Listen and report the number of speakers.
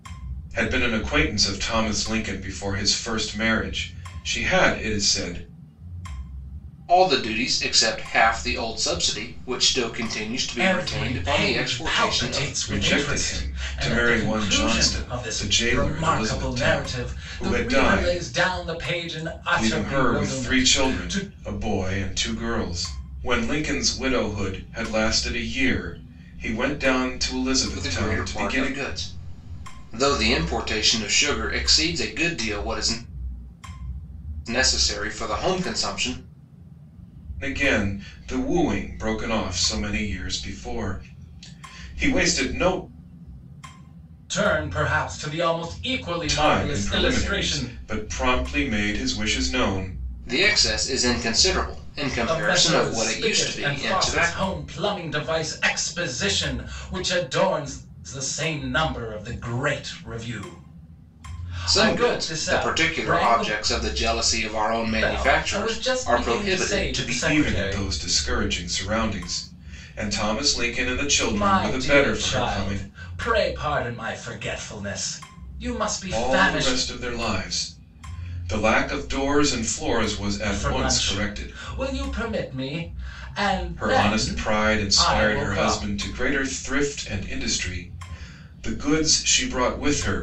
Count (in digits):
3